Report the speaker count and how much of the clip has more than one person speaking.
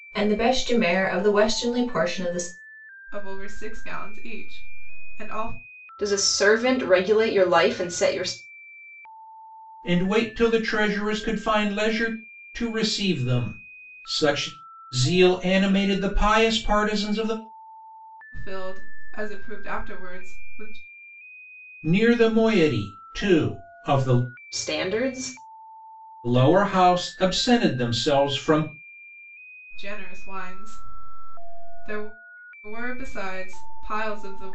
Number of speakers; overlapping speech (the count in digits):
4, no overlap